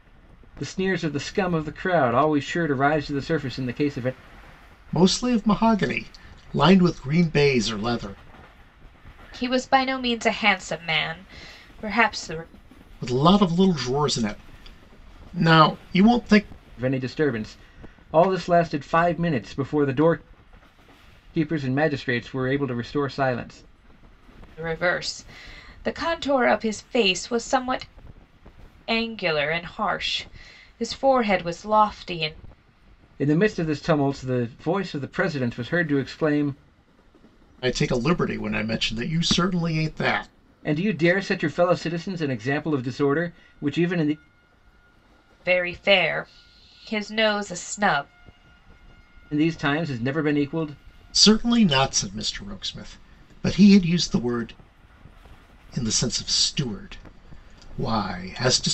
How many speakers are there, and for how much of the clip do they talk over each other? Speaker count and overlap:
3, no overlap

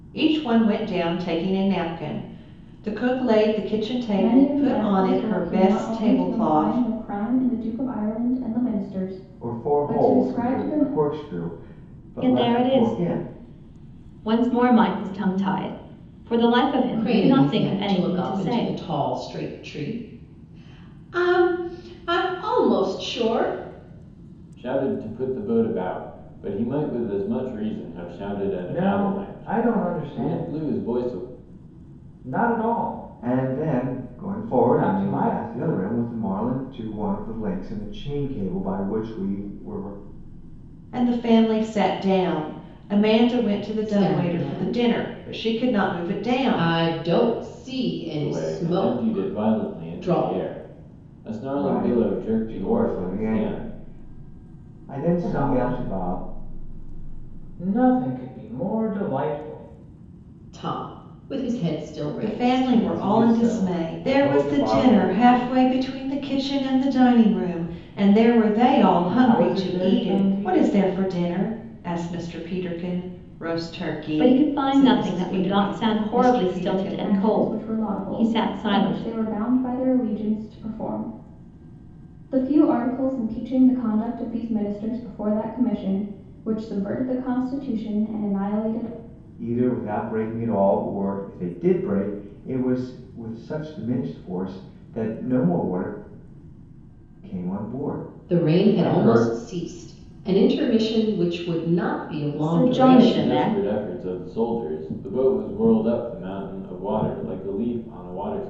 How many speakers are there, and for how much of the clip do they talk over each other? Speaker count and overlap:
7, about 30%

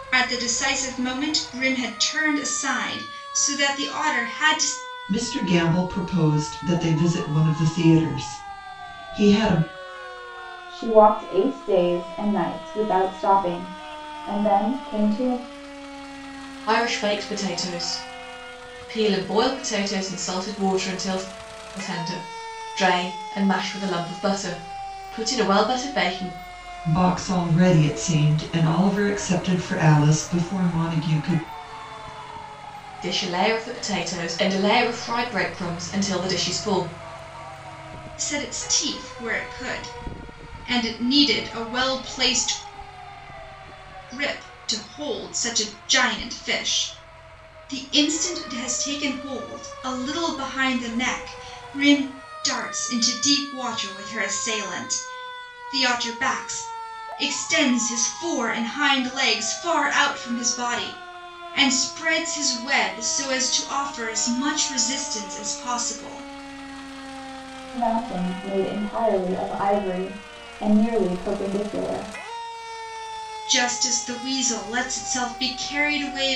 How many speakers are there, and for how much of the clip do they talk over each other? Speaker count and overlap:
4, no overlap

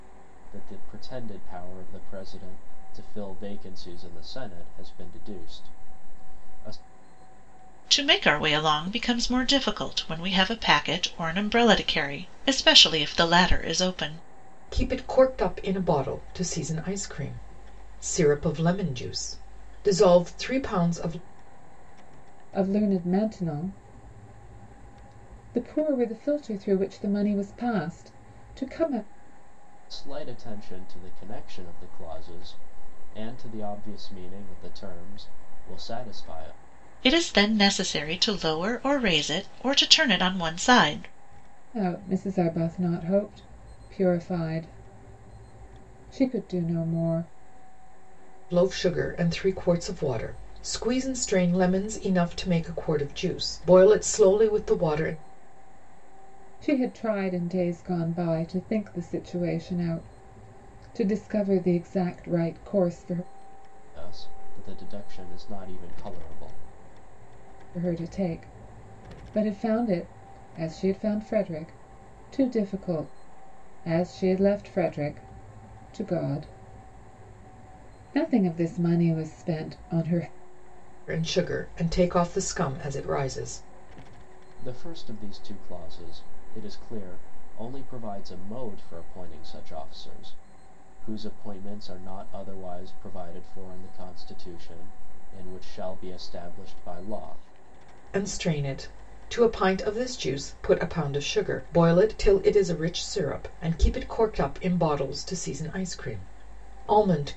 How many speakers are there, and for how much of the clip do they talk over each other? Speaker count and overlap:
4, no overlap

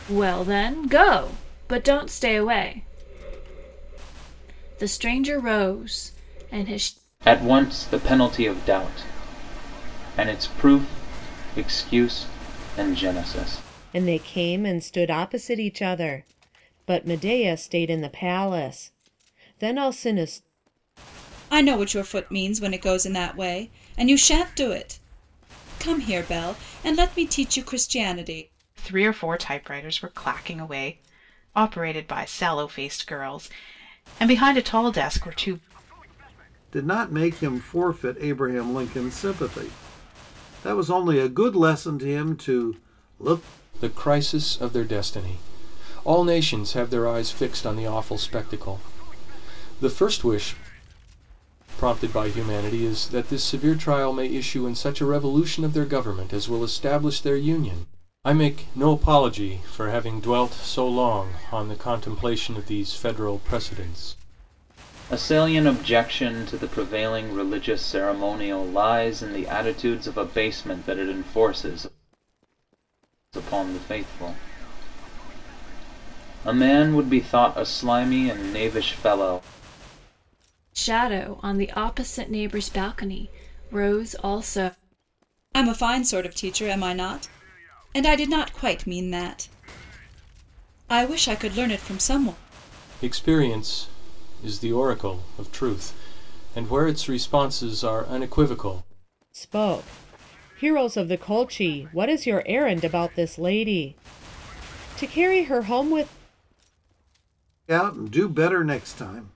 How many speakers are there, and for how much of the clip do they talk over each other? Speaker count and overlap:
7, no overlap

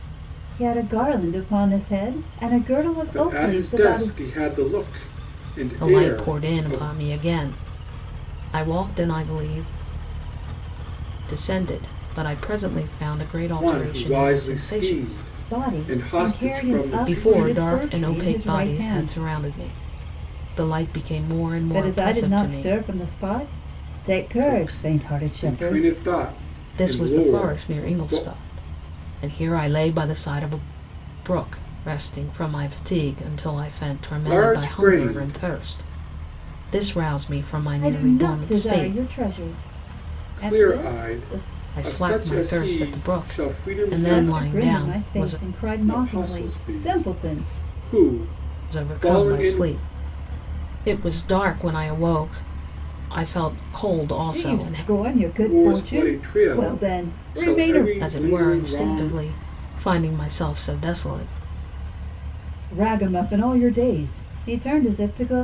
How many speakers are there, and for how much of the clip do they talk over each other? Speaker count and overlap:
3, about 40%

